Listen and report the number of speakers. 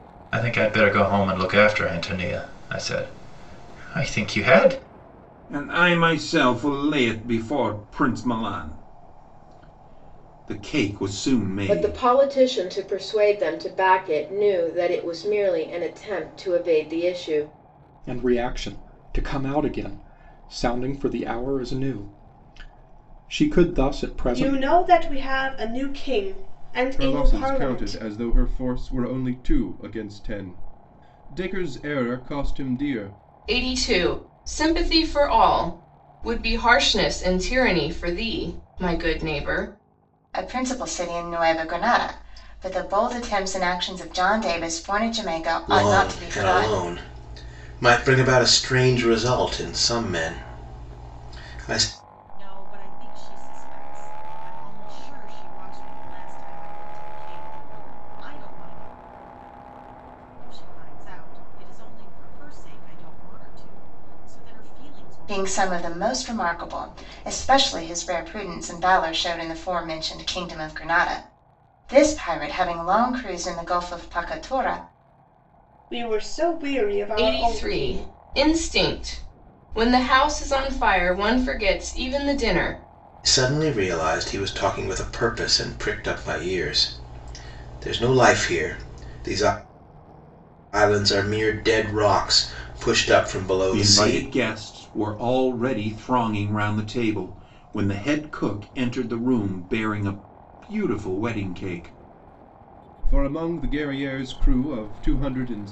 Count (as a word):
ten